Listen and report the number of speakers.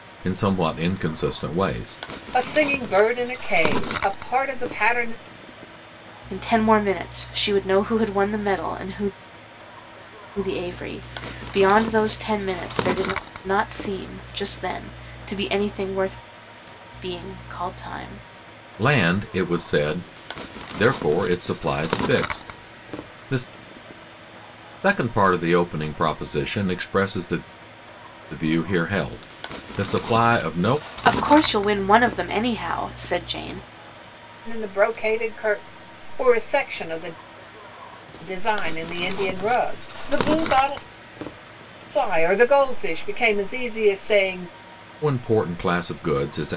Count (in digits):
3